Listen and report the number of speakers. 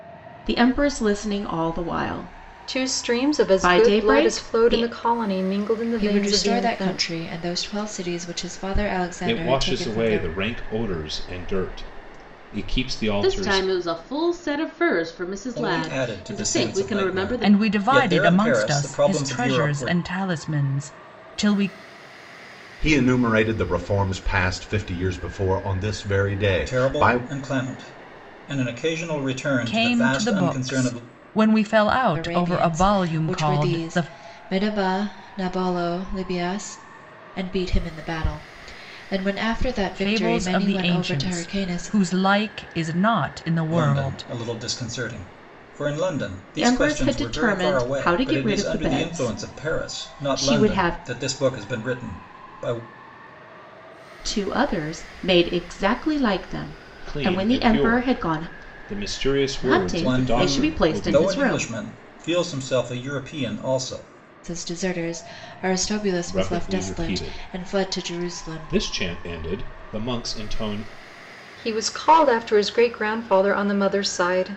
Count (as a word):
eight